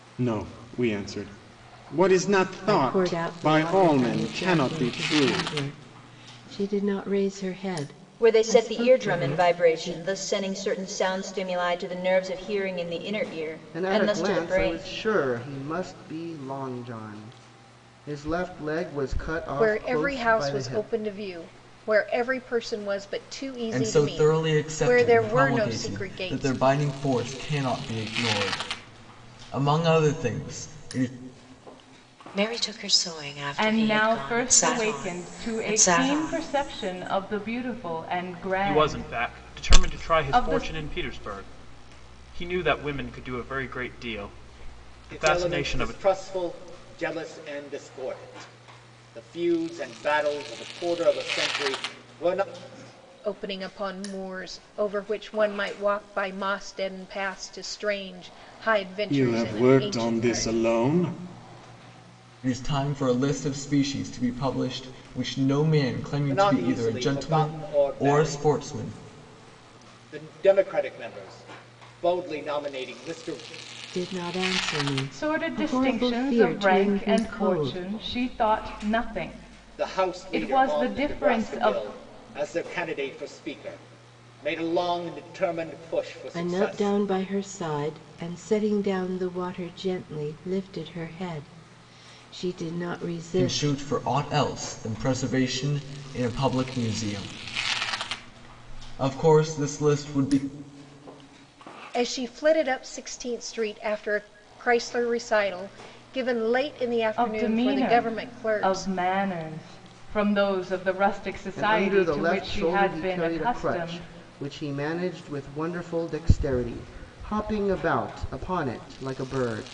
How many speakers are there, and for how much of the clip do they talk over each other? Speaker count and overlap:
ten, about 26%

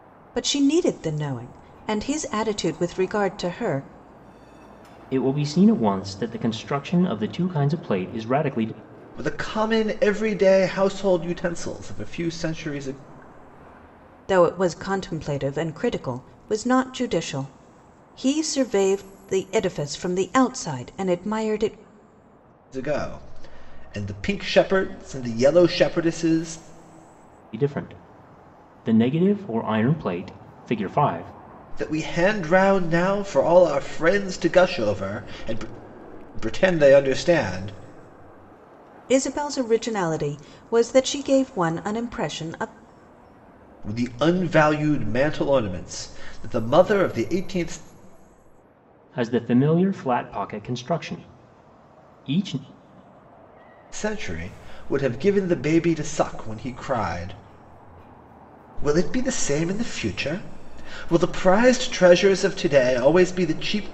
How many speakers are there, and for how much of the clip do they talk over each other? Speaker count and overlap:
three, no overlap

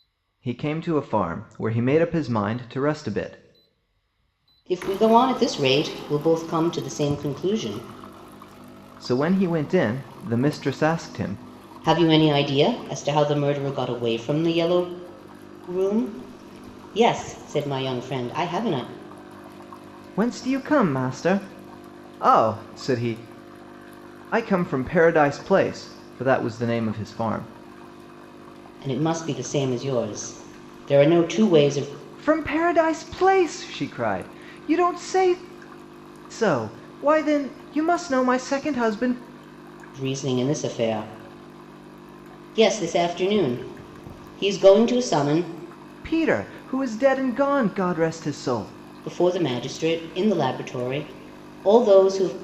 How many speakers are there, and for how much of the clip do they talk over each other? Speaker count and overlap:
two, no overlap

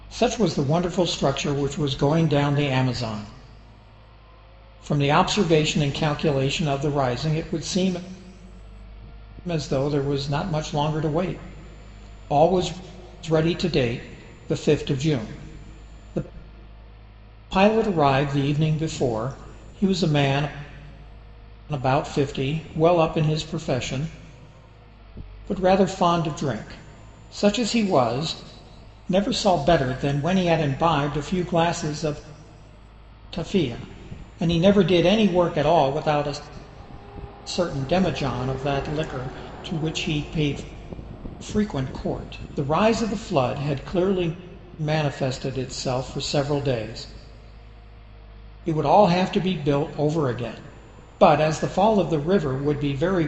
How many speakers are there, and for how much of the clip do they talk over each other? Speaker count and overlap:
one, no overlap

